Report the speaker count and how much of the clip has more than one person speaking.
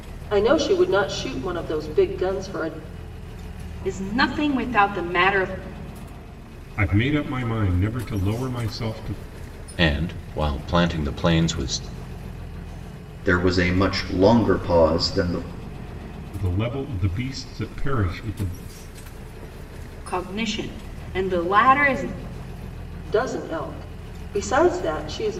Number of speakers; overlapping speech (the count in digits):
5, no overlap